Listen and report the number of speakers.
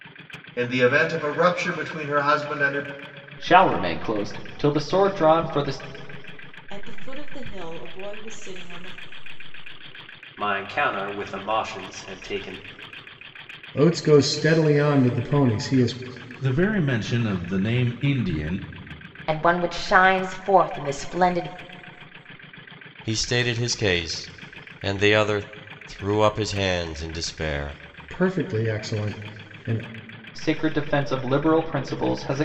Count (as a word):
eight